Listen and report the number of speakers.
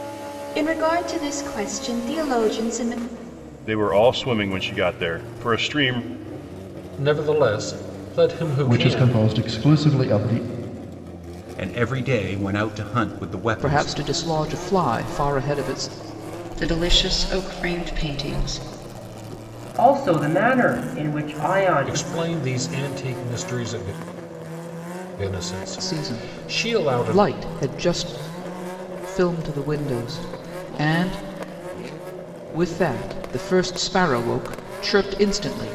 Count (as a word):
eight